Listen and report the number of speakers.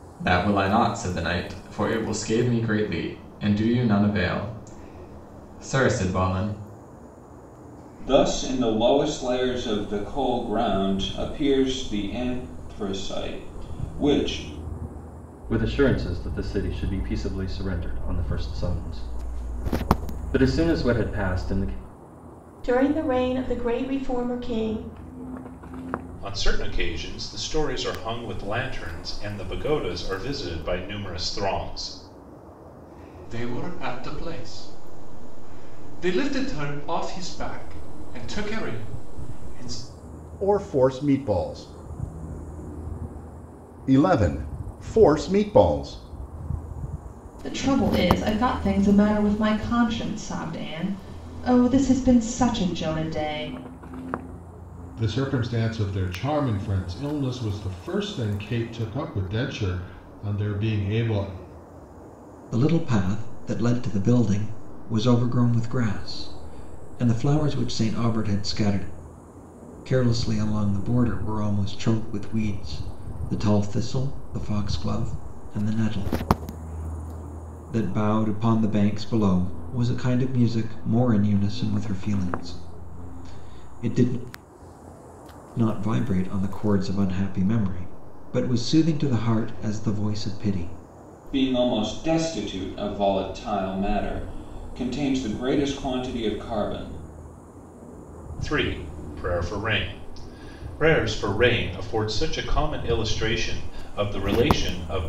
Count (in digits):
10